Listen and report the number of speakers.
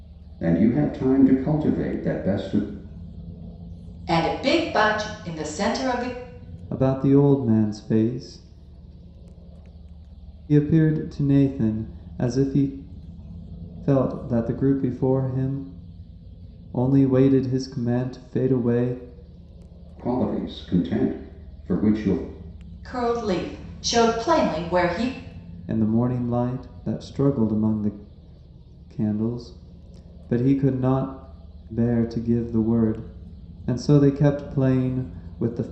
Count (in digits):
3